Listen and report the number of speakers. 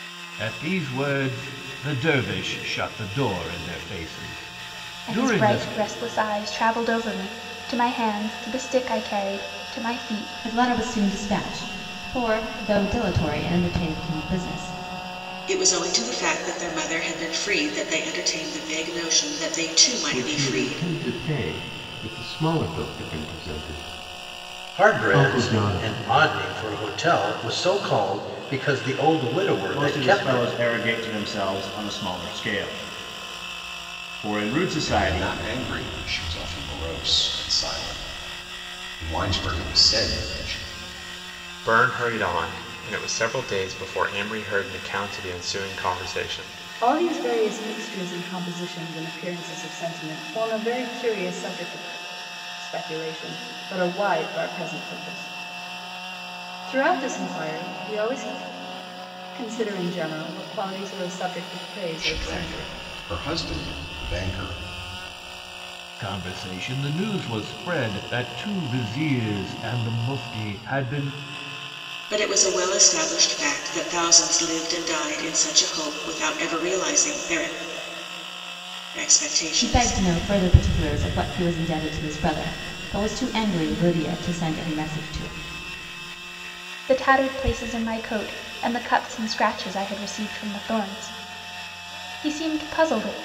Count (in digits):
10